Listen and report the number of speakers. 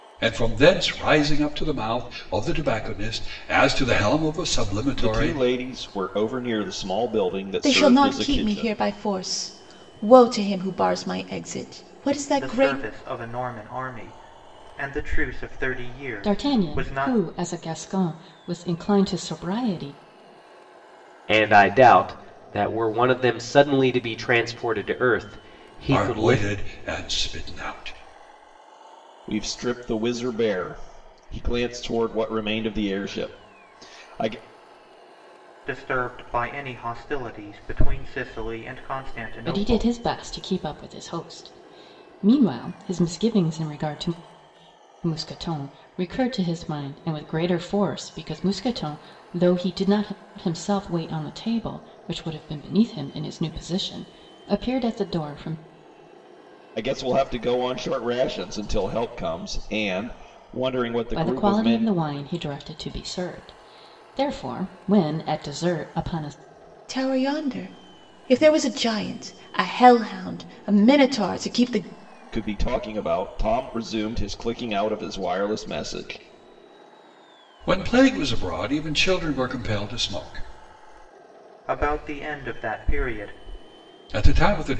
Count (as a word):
six